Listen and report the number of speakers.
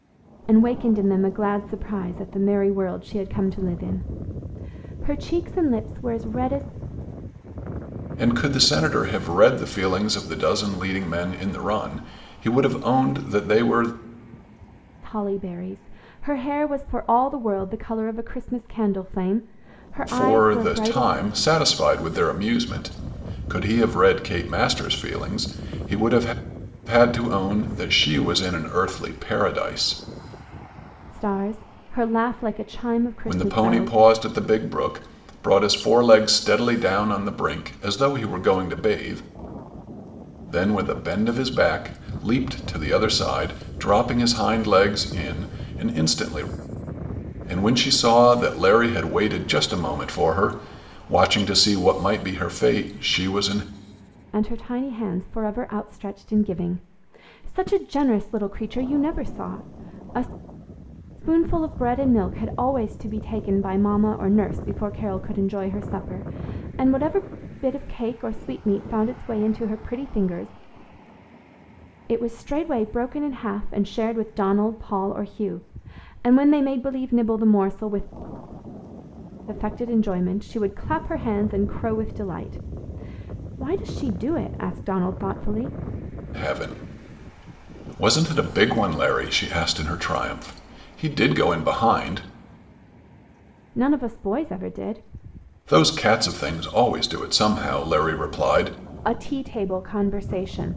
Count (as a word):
two